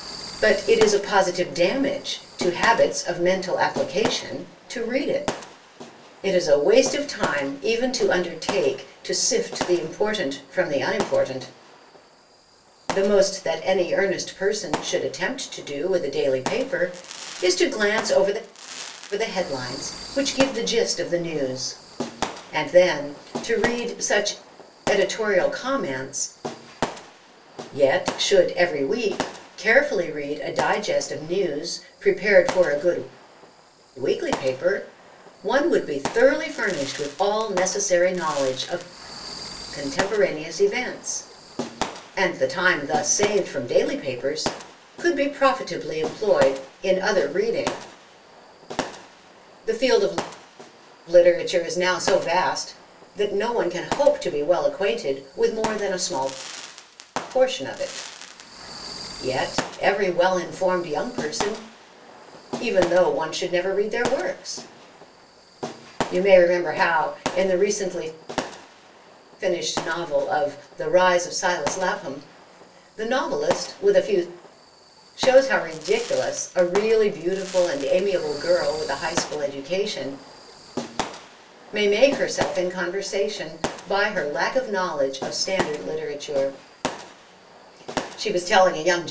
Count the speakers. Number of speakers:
1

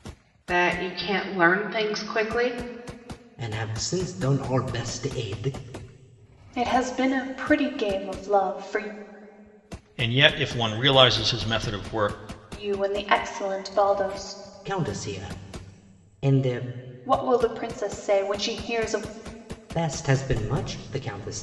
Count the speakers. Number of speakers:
4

